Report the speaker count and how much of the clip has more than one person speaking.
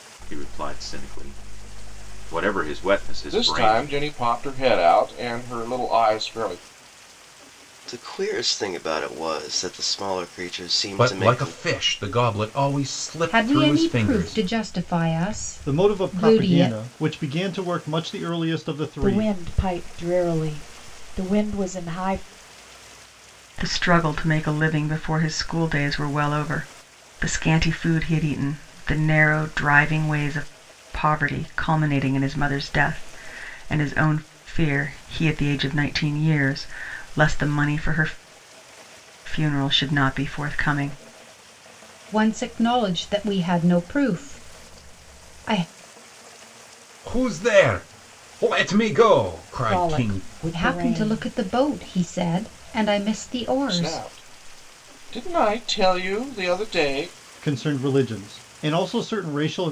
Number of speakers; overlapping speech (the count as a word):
eight, about 10%